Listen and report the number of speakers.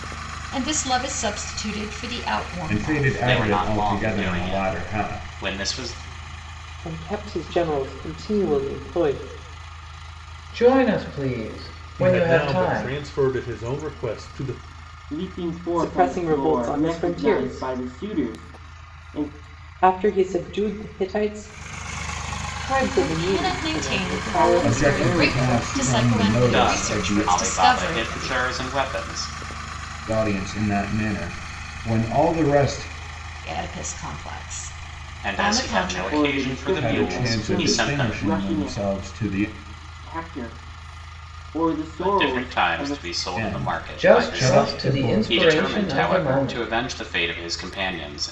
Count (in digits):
7